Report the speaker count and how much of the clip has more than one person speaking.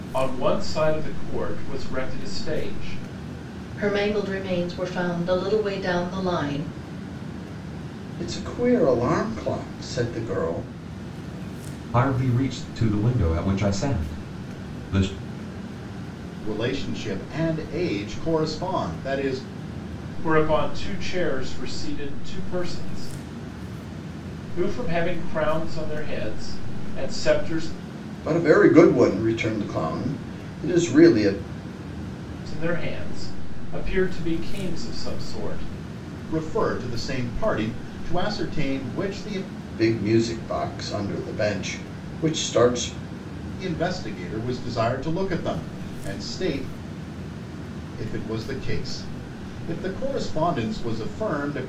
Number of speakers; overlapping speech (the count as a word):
five, no overlap